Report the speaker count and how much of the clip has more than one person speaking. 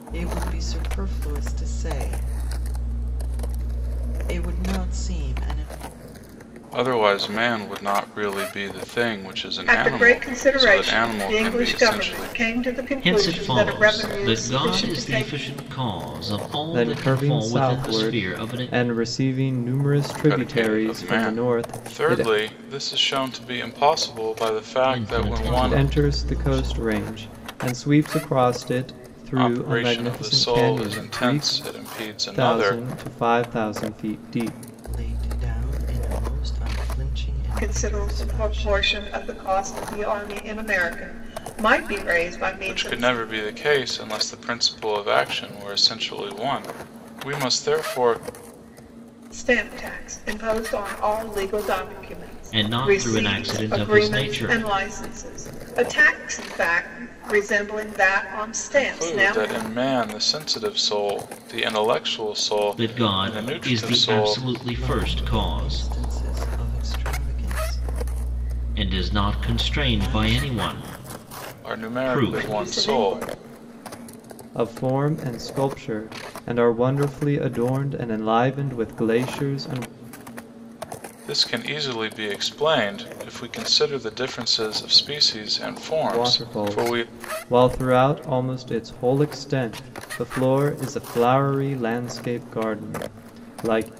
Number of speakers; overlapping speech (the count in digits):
5, about 28%